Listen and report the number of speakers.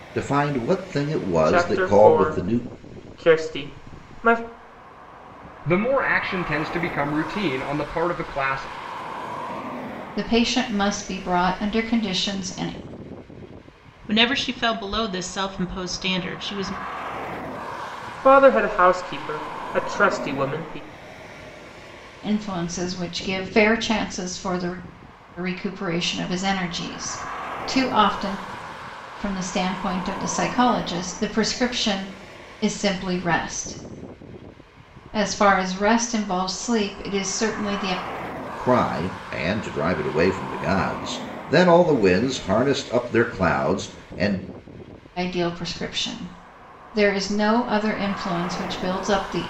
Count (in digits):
5